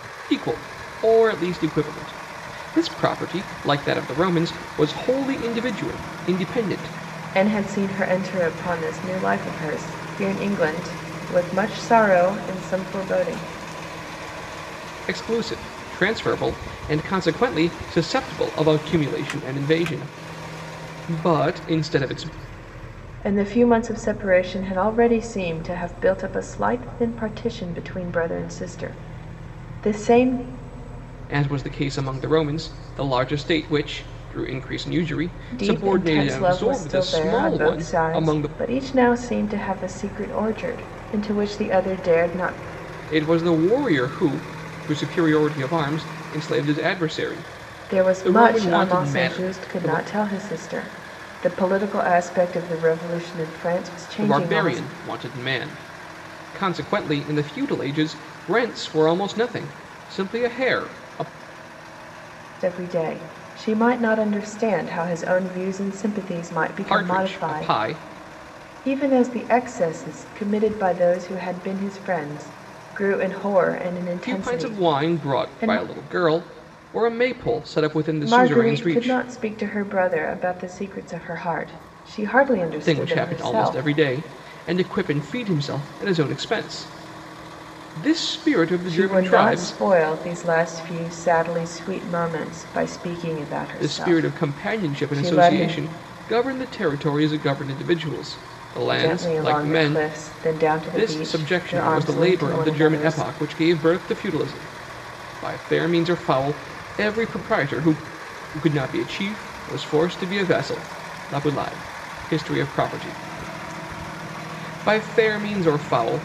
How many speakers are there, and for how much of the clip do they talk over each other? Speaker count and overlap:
2, about 15%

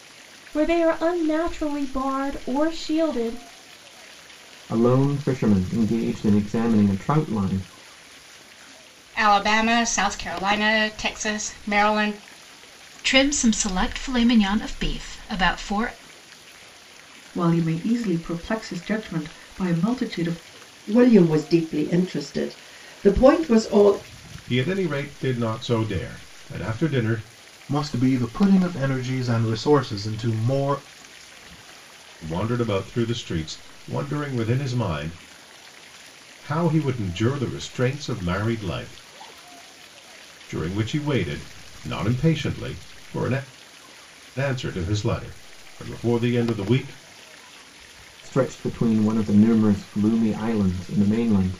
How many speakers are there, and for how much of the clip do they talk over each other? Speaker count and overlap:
8, no overlap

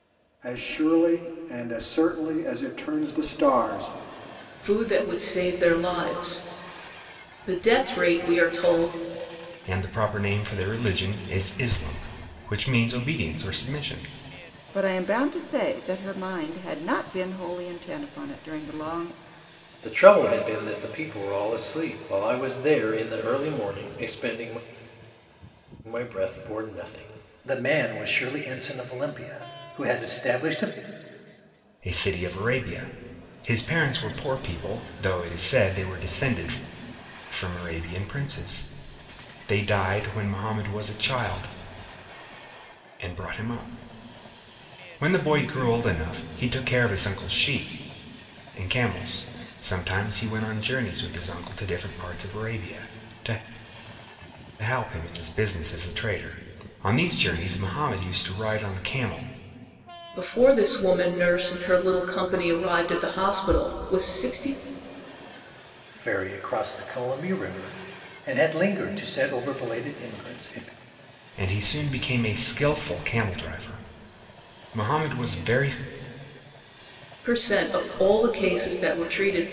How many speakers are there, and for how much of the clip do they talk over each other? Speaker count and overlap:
5, no overlap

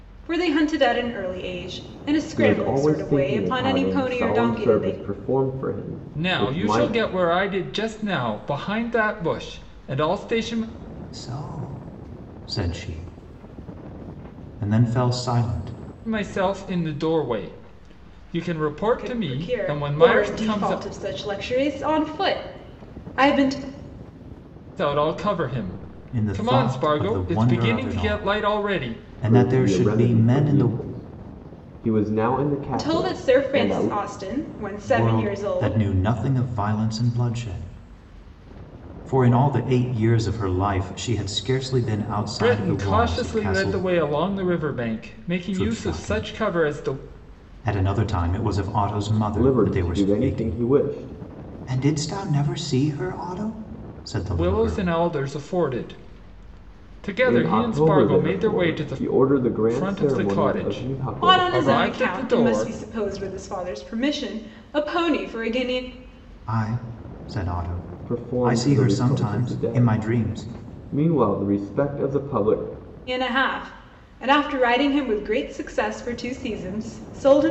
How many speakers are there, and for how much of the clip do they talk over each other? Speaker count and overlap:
4, about 32%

